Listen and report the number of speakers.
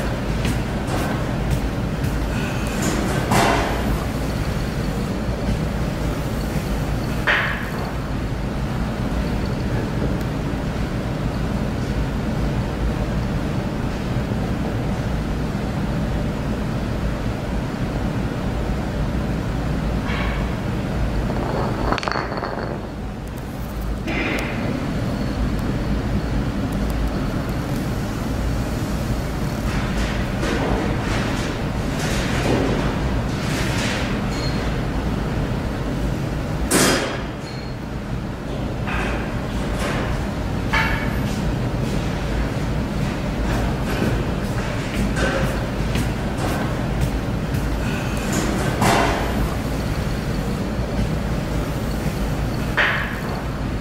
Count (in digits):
0